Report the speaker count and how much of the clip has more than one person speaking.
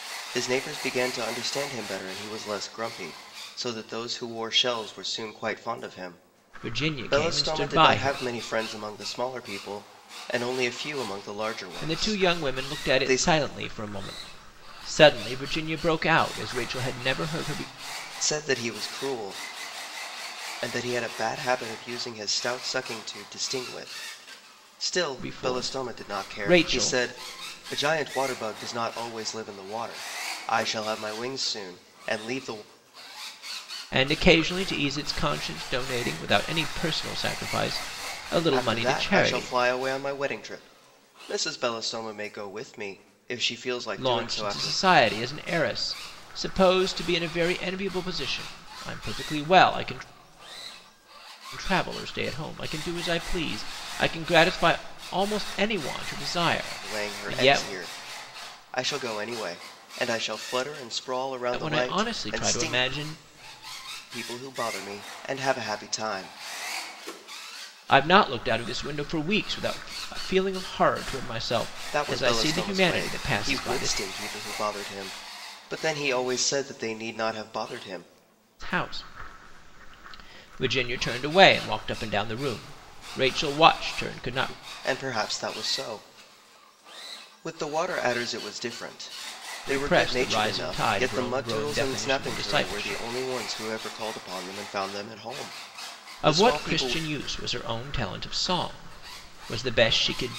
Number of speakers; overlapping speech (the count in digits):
2, about 15%